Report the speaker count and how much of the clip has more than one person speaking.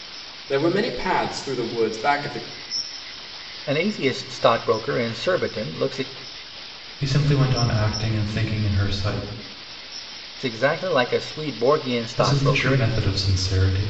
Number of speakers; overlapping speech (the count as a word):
three, about 5%